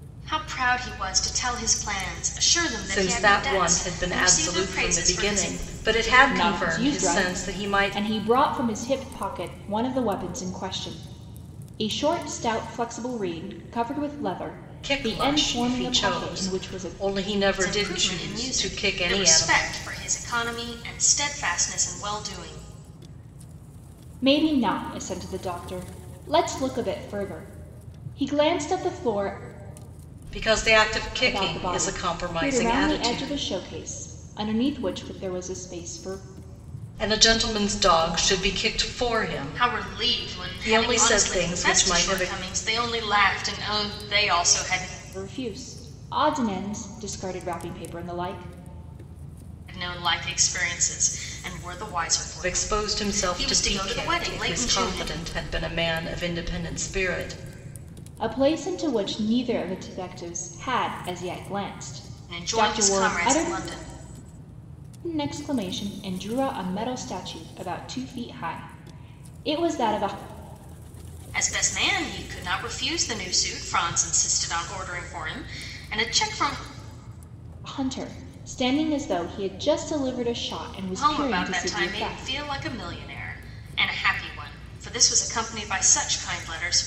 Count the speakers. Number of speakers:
3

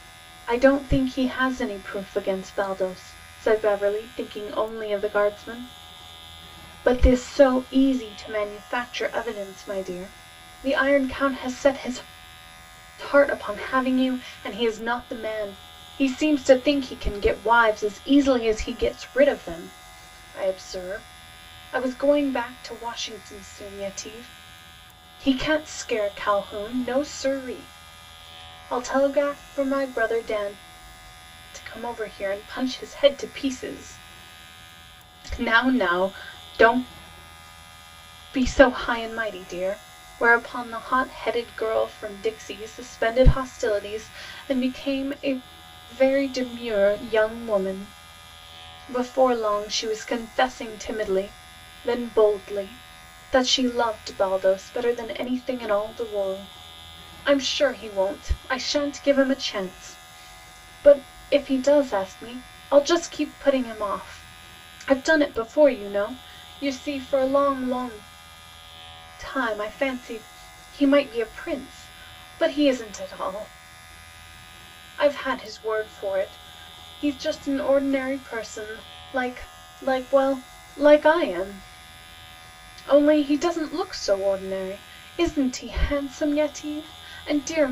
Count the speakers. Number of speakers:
1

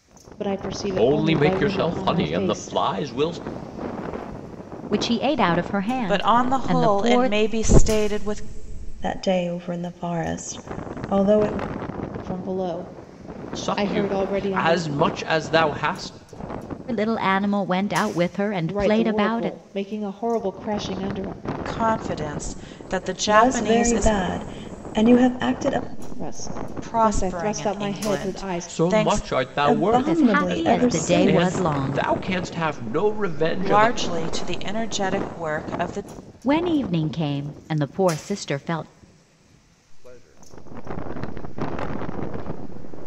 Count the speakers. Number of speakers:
6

